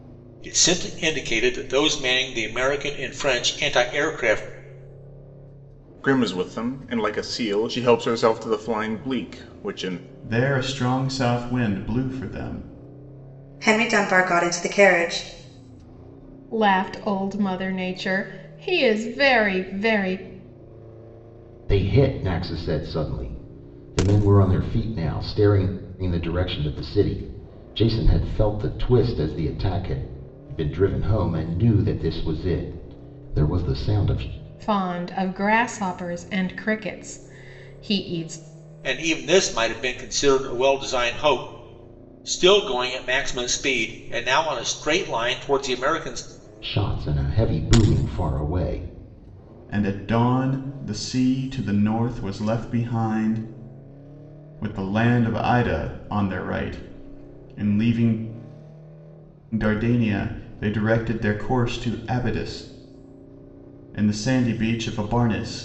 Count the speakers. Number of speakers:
6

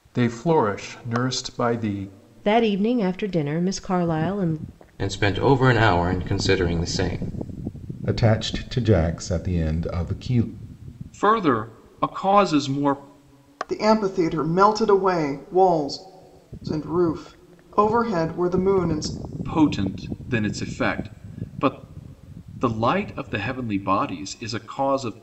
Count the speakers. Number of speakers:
6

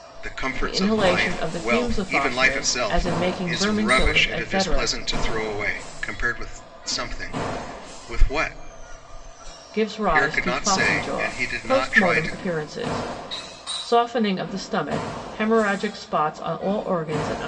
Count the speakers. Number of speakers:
2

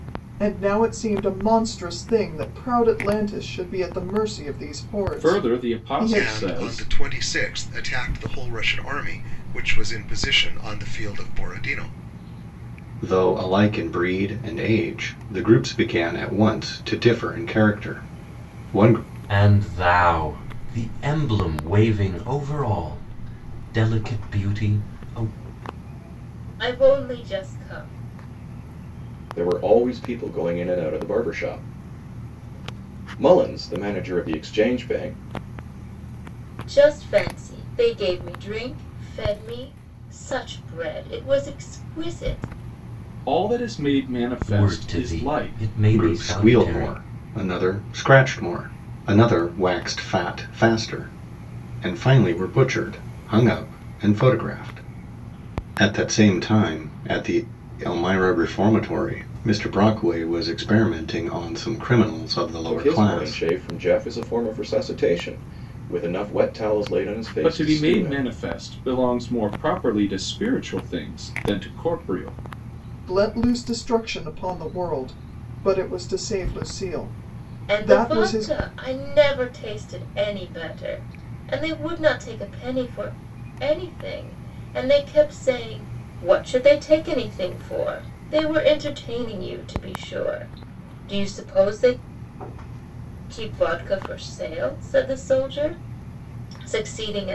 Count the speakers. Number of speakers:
7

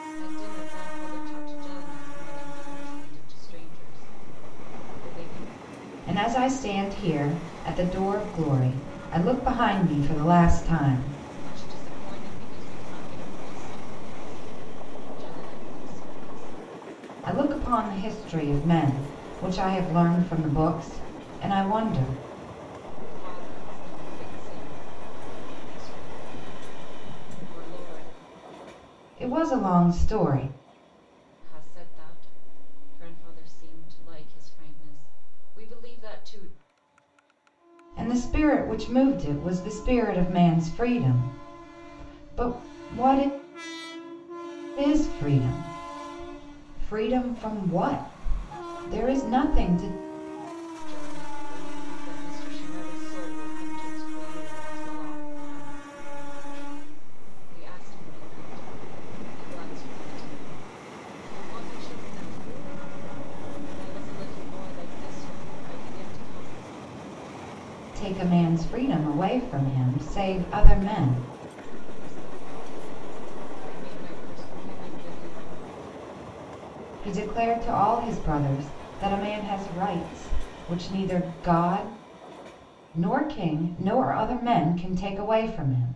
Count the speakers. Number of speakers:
2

